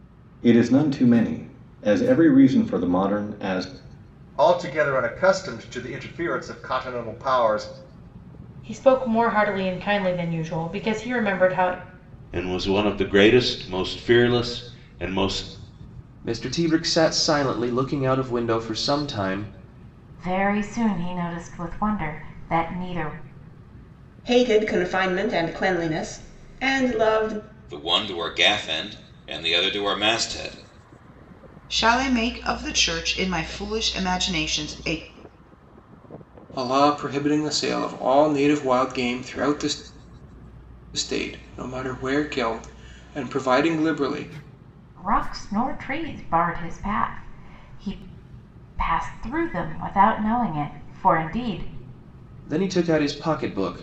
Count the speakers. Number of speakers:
10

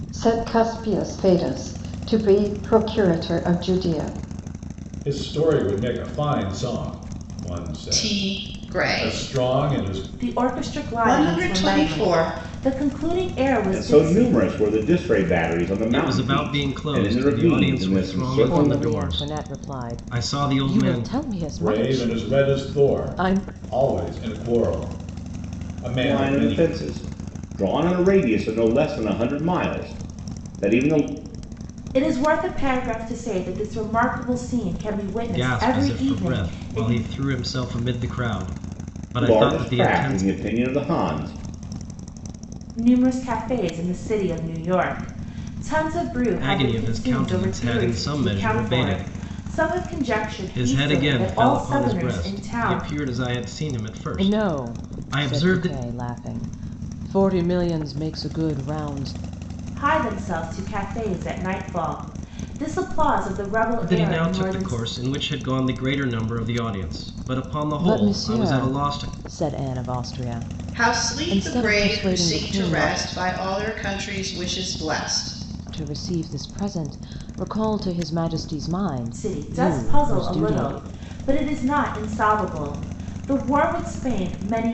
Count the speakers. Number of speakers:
7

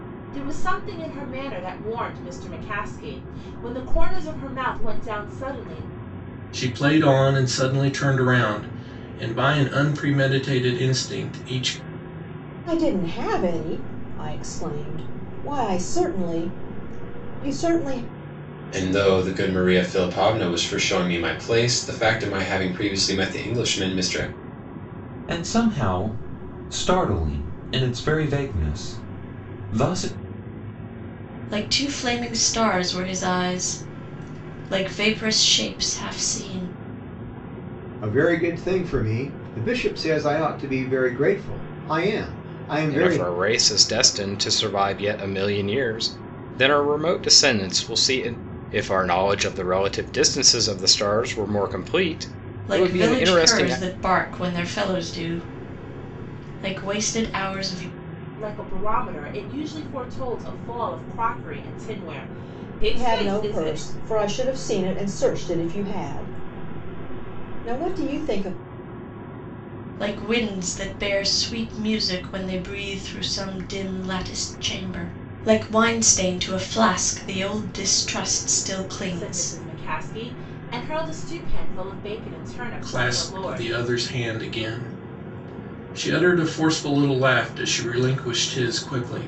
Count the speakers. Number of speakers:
8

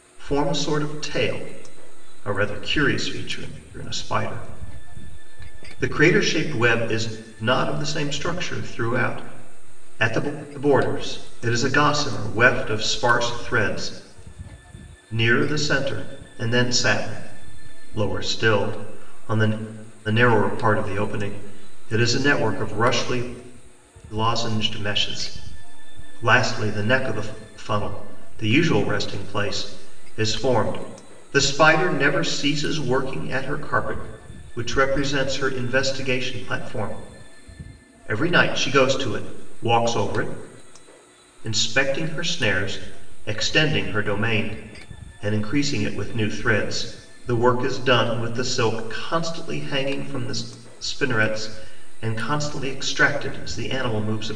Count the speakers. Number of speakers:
1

